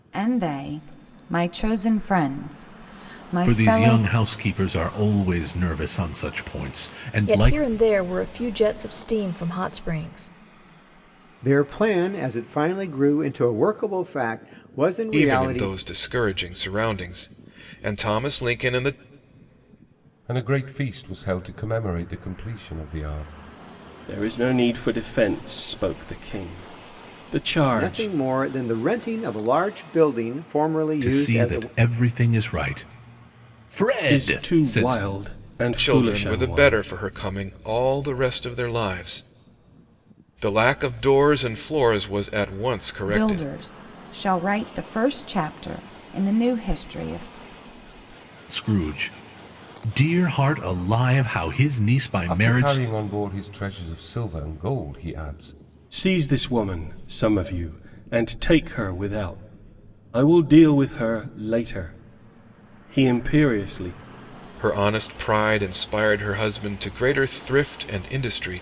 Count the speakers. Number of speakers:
seven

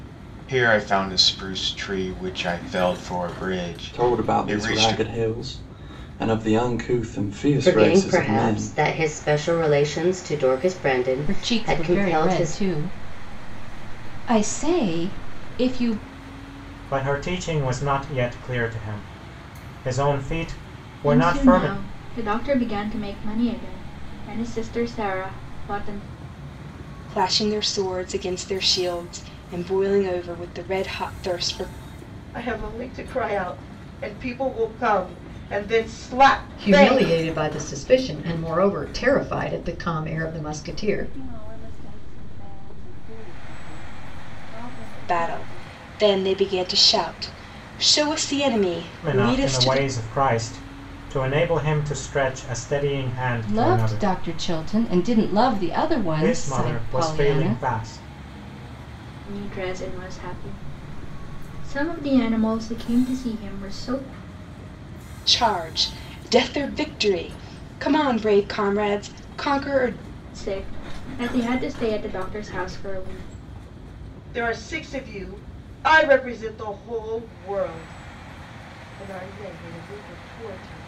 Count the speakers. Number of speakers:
ten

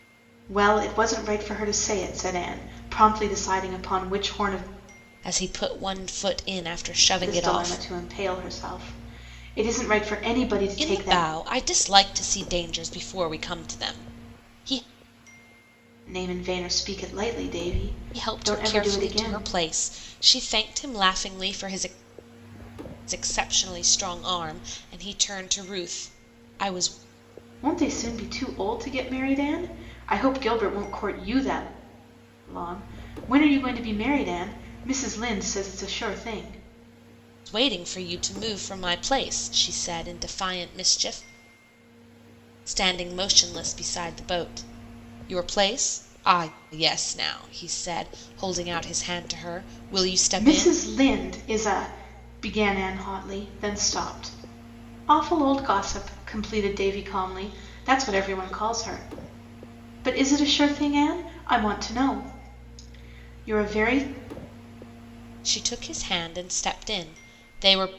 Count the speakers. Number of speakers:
two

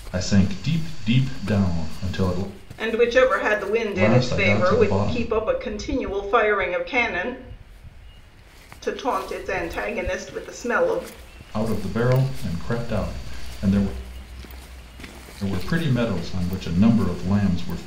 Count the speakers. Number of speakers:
two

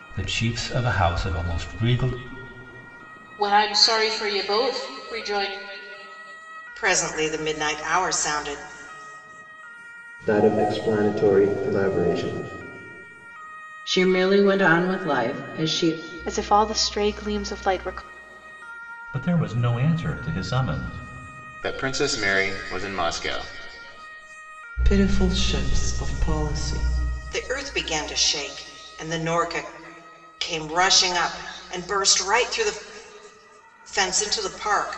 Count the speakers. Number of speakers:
nine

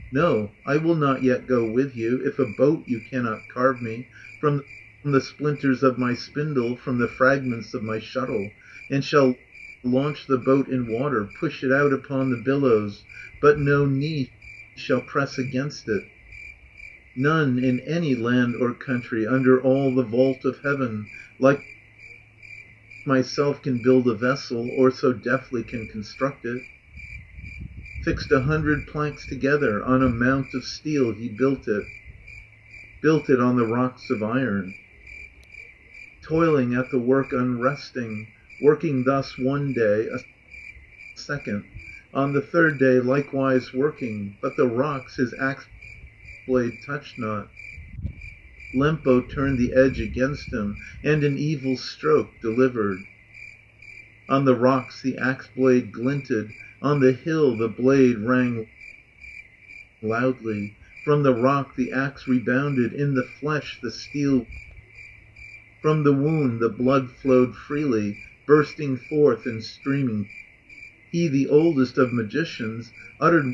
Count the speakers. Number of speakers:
one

